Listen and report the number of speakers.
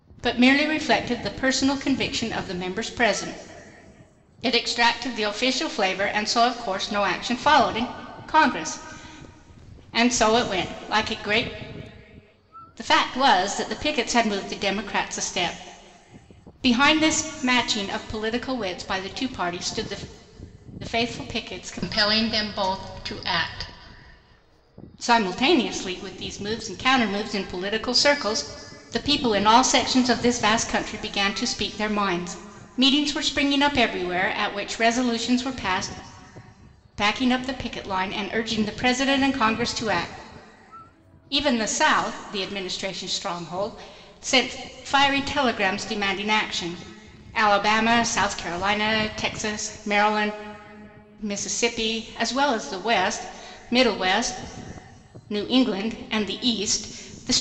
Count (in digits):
1